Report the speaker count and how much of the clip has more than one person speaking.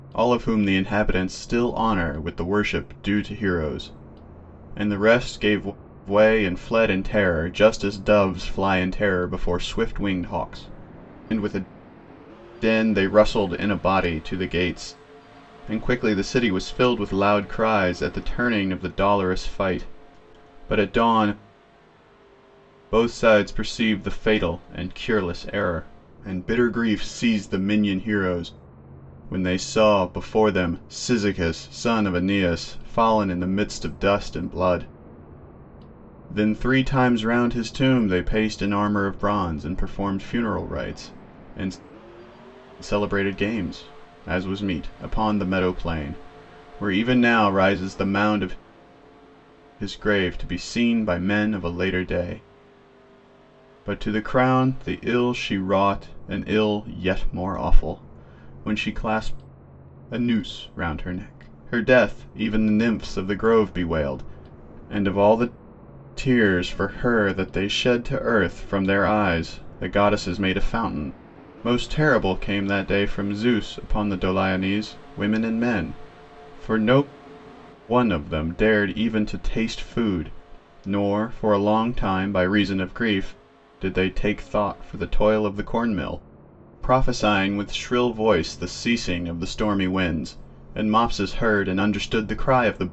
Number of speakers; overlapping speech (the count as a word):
one, no overlap